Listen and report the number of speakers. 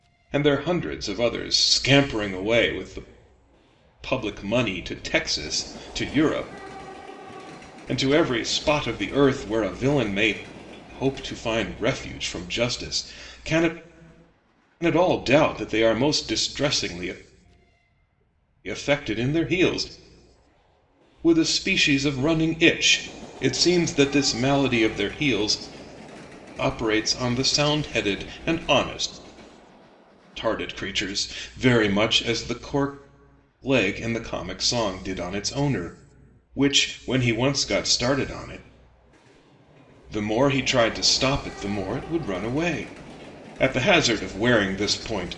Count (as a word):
one